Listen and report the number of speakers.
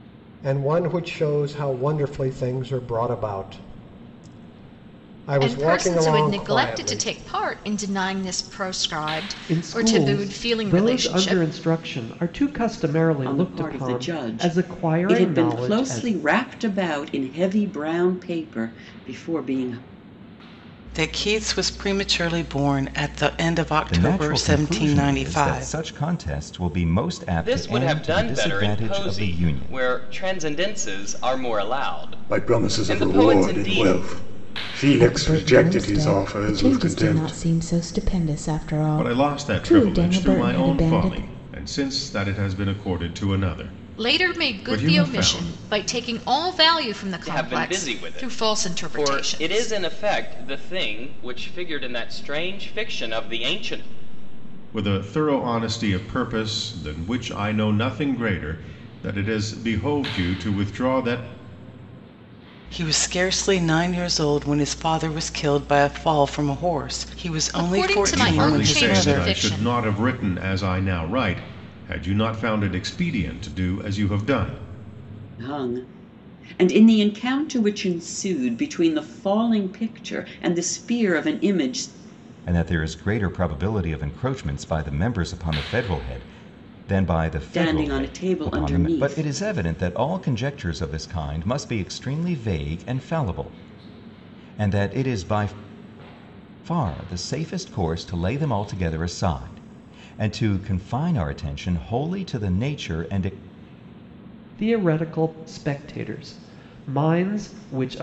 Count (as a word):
ten